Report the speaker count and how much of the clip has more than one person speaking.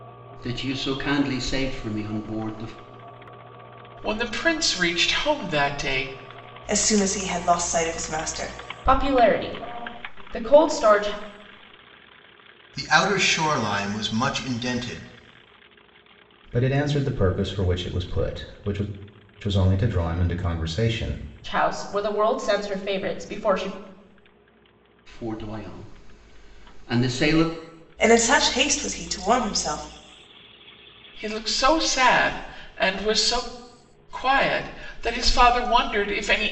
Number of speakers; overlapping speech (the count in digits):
6, no overlap